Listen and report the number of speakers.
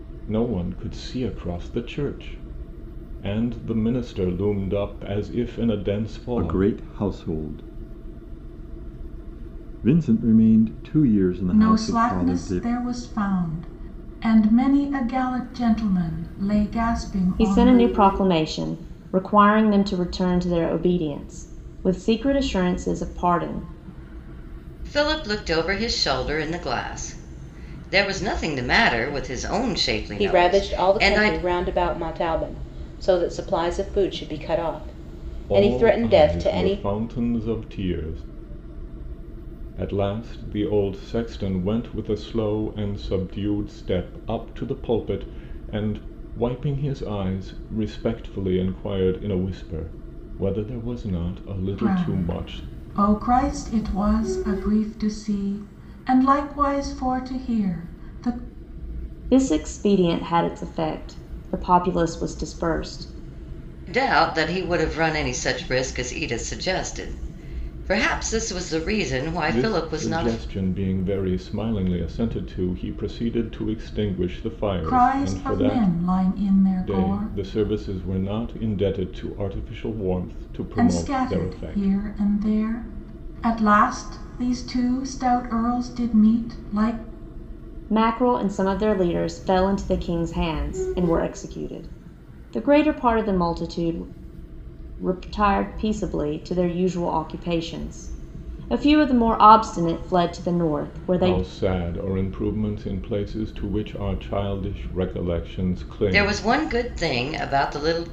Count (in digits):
6